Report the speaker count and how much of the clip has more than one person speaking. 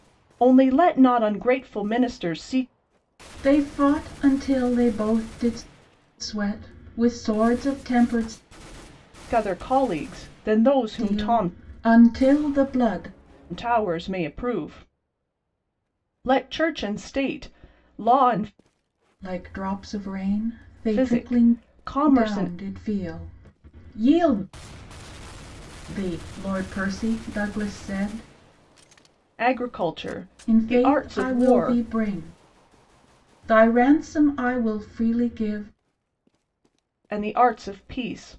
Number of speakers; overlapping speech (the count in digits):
2, about 9%